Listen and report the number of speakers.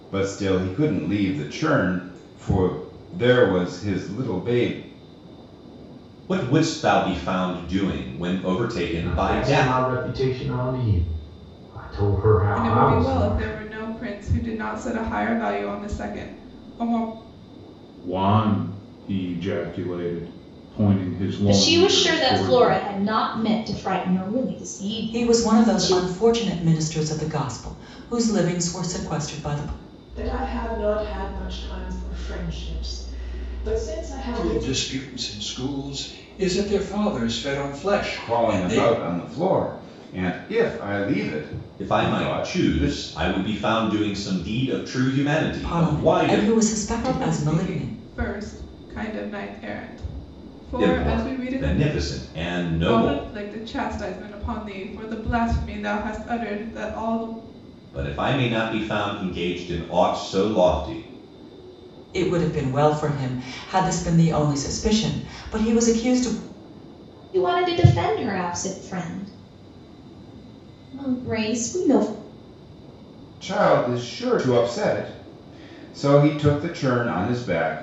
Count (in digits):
9